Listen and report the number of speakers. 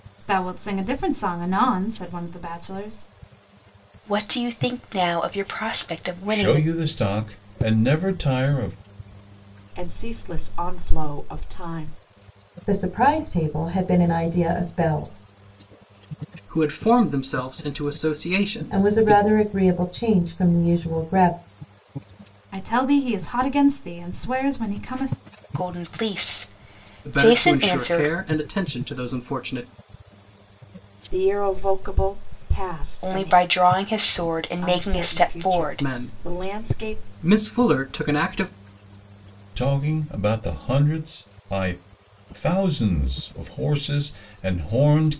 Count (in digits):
6